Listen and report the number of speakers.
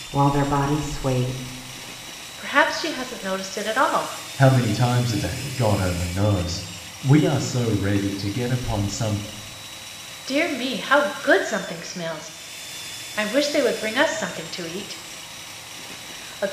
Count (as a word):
three